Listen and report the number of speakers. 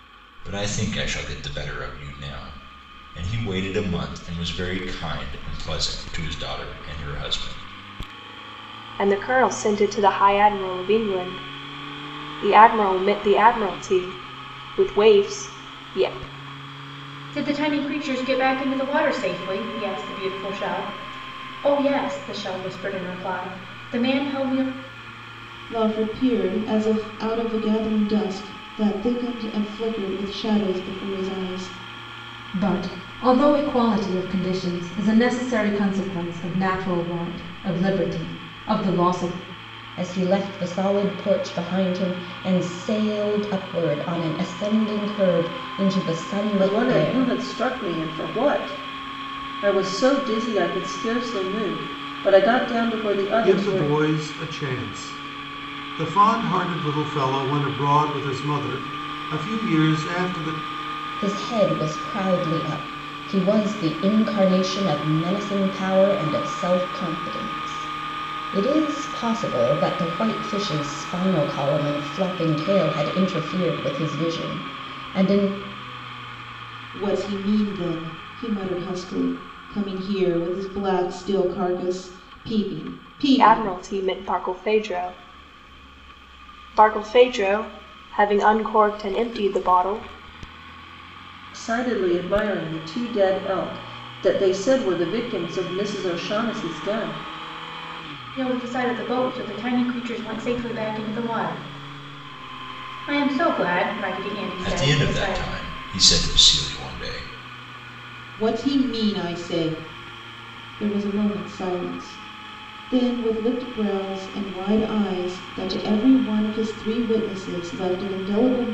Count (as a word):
eight